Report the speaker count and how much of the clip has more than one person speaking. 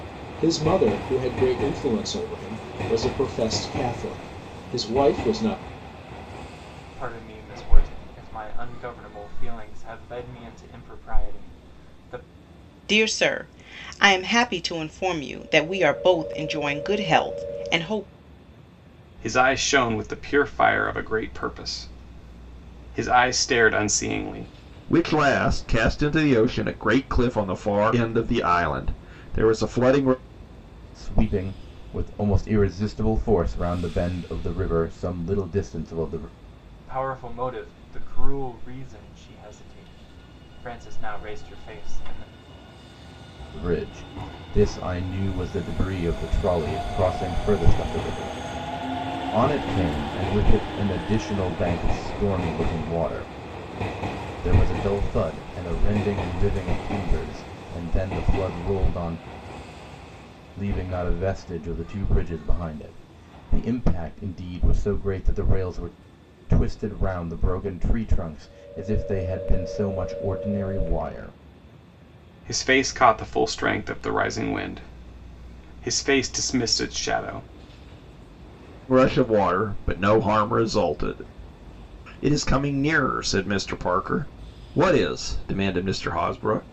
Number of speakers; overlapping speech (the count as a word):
six, no overlap